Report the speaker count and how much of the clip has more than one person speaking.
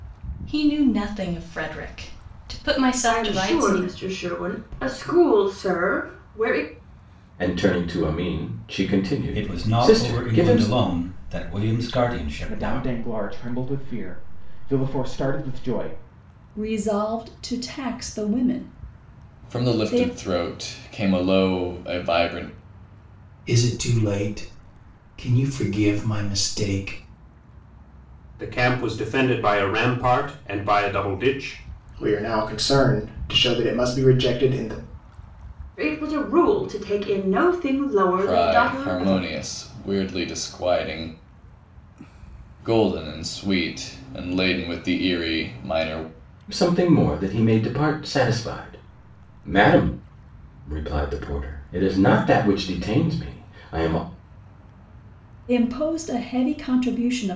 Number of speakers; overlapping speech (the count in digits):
10, about 8%